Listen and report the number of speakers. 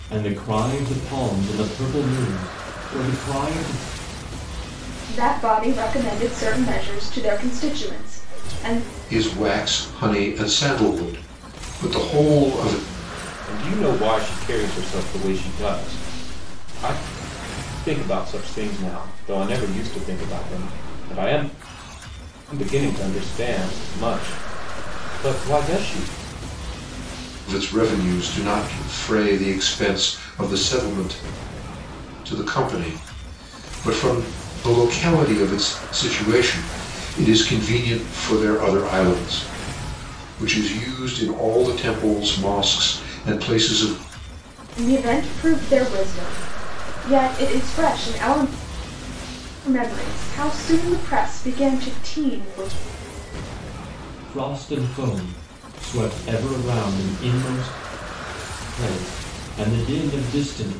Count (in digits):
4